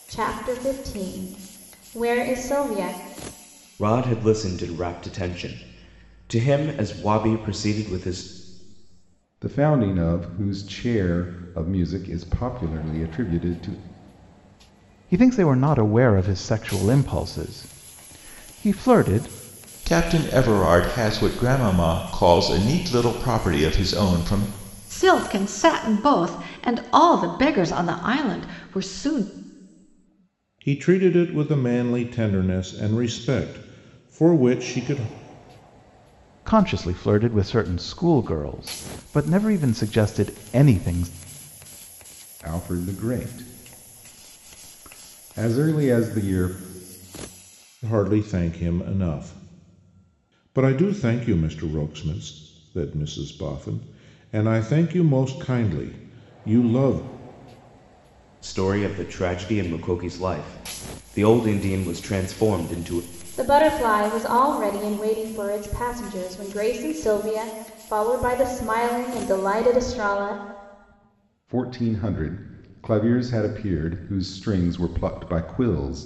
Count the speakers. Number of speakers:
7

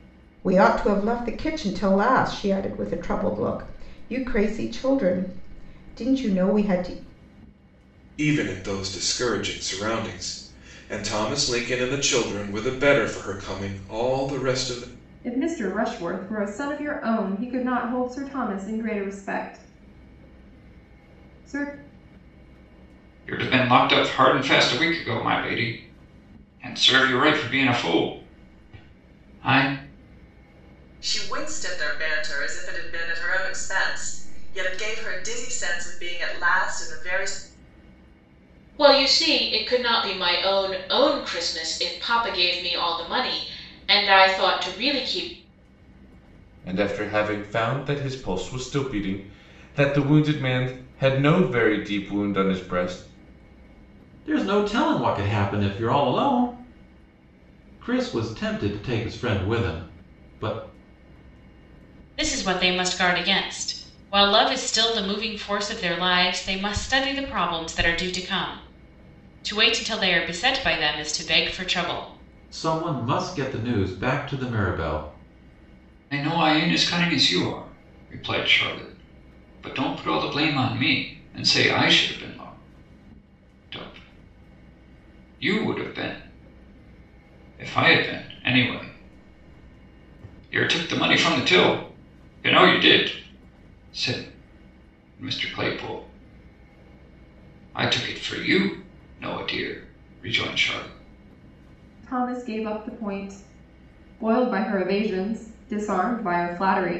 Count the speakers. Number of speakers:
9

